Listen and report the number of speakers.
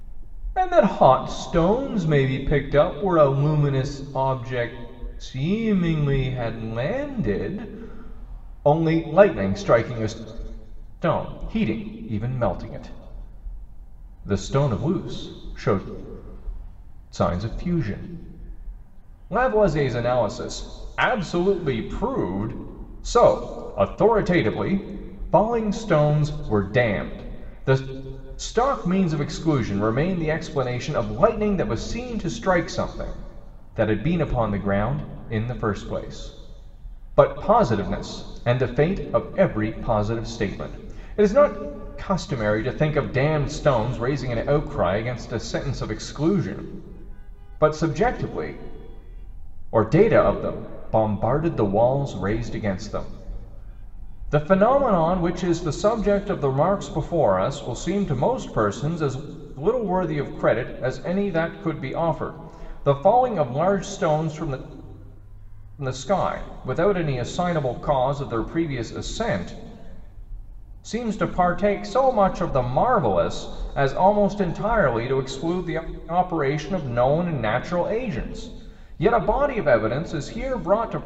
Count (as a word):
one